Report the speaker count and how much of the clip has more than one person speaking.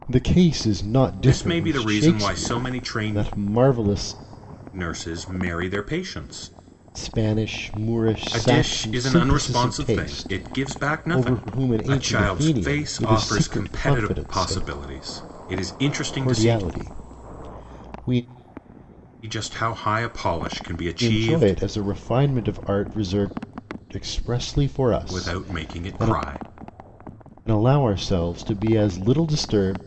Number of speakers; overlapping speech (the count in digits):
2, about 36%